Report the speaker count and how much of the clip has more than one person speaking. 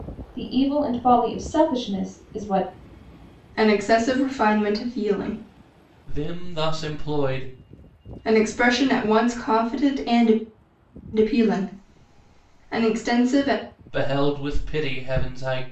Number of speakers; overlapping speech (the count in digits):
3, no overlap